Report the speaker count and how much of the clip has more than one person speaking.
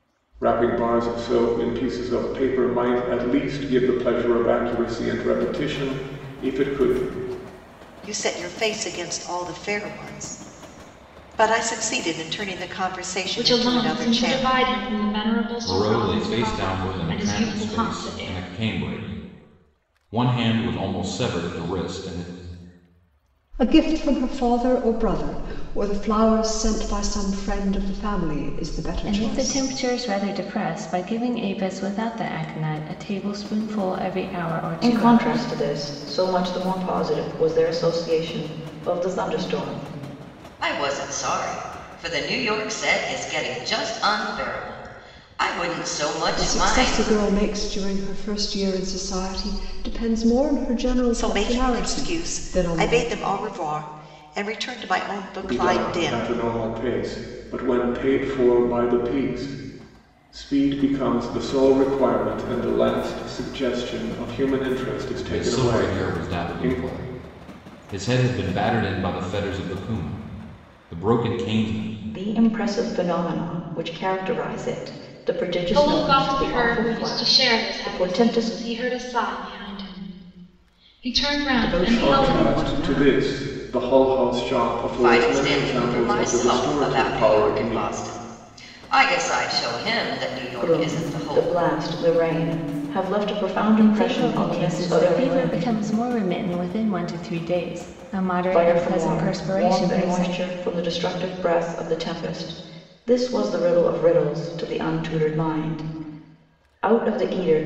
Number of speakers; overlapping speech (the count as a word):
eight, about 21%